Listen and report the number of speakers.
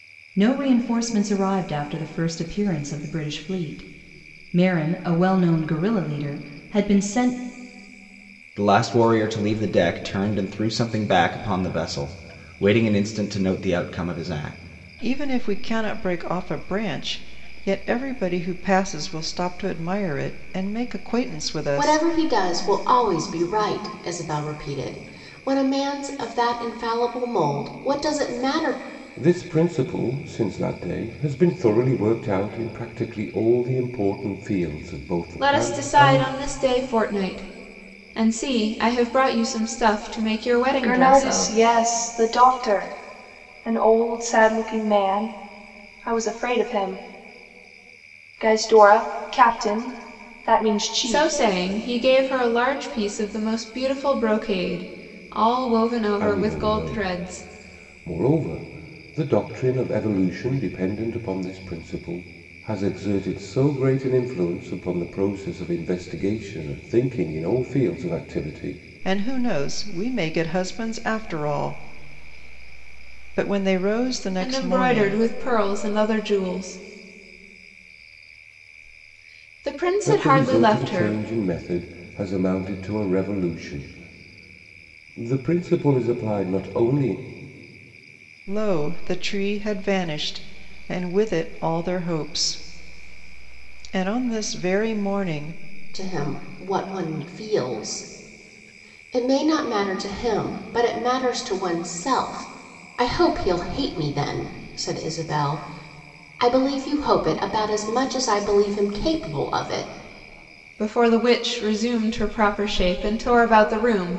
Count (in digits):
7